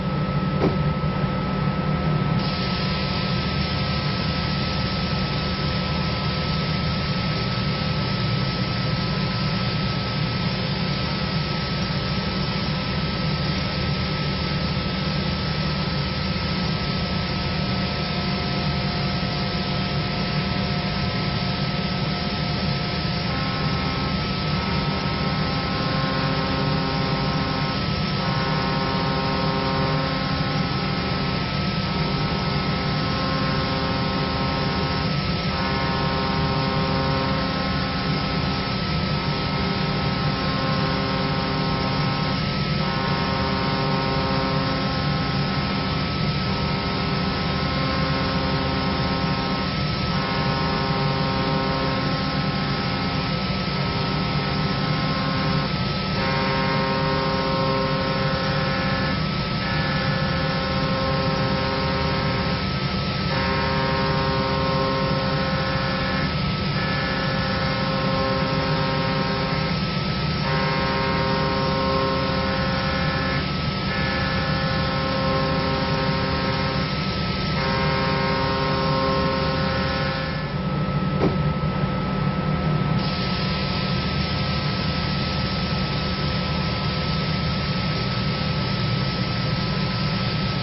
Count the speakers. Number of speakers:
0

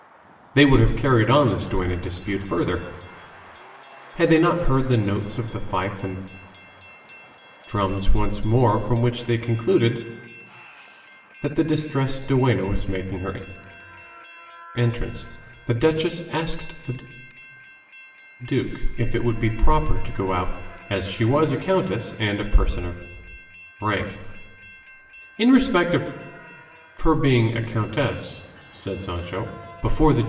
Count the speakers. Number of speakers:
1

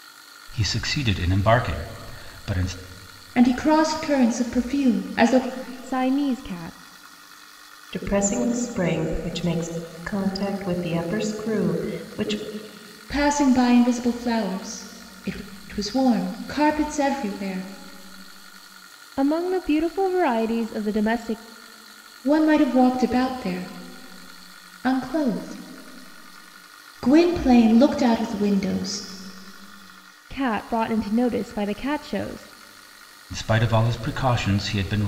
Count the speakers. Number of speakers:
4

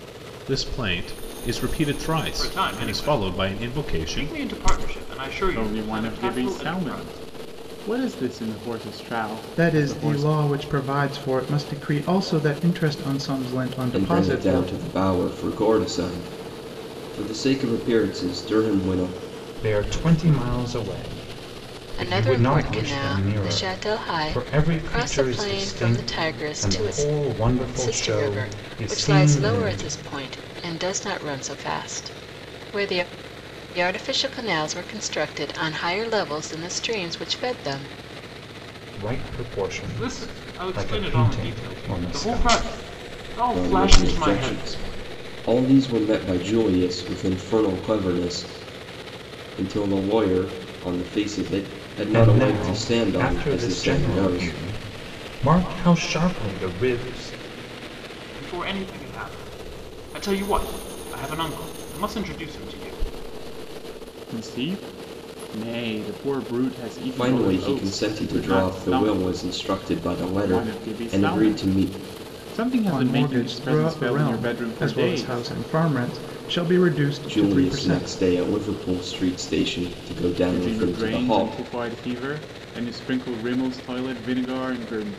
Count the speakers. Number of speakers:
7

